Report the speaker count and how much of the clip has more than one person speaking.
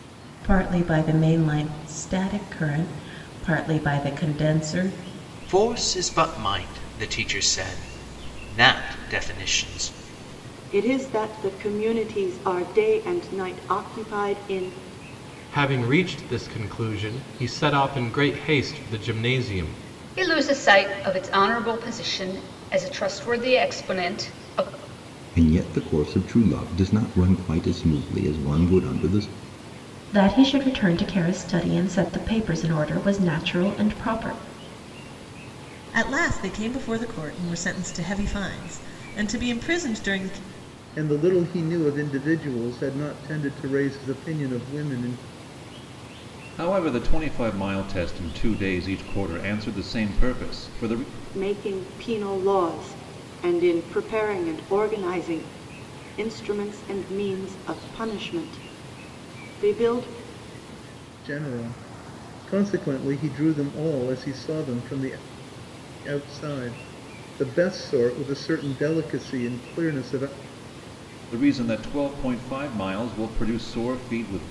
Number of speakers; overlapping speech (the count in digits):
10, no overlap